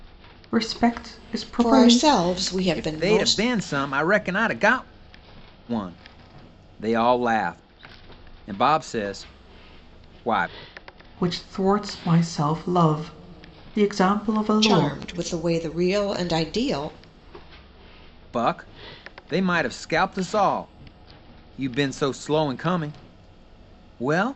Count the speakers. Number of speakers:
3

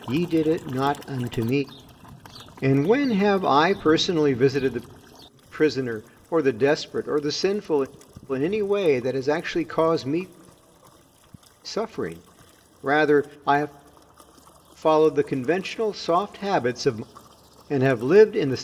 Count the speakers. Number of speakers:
1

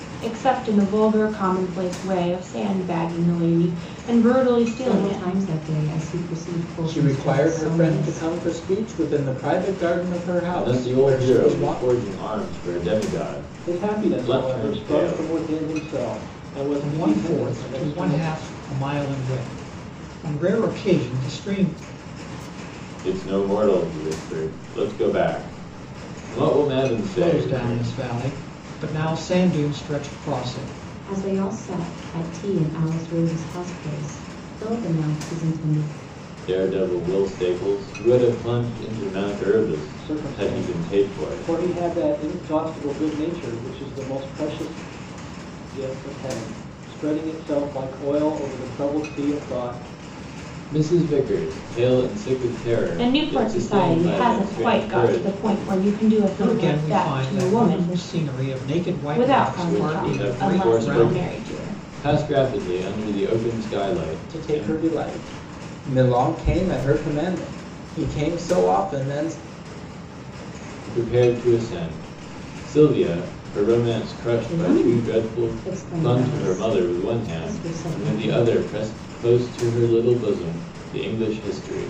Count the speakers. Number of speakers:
6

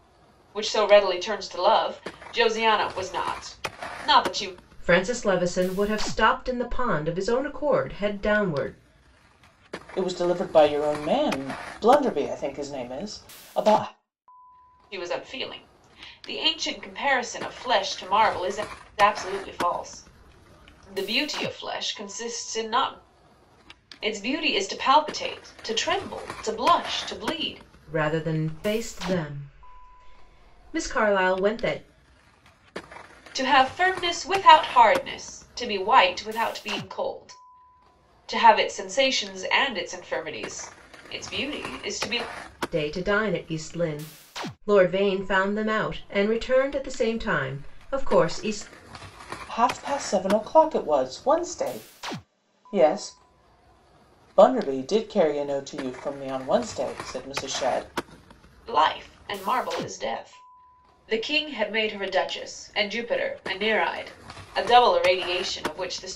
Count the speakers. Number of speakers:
3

